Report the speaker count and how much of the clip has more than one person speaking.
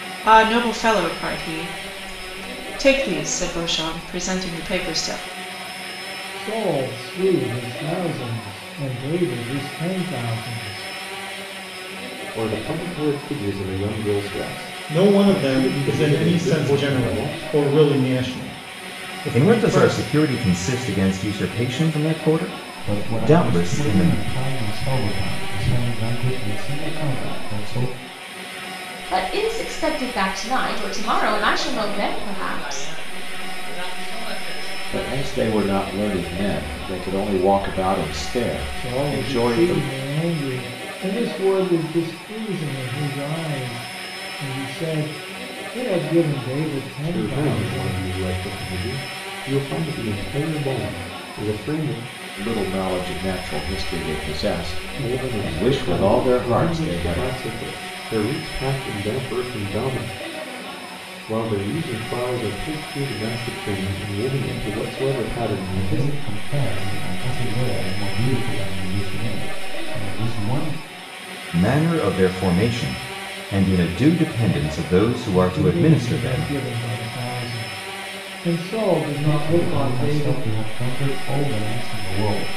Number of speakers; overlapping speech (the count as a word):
nine, about 18%